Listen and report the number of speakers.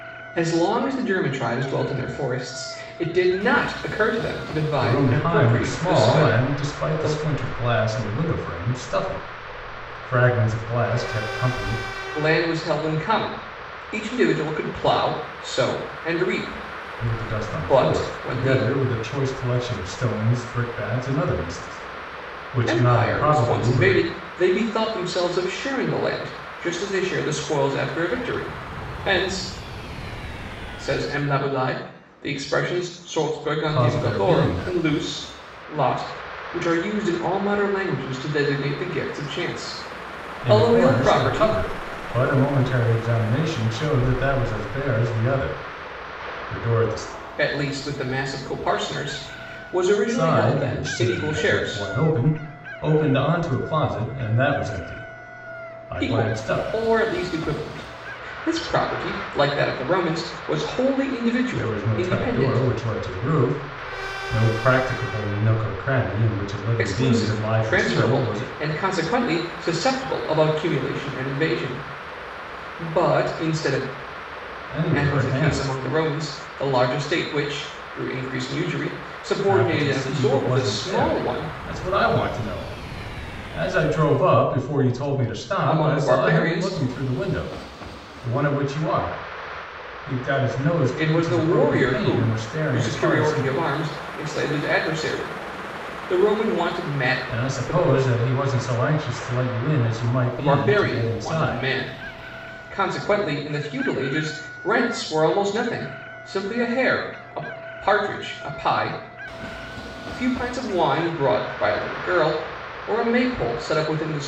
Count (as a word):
two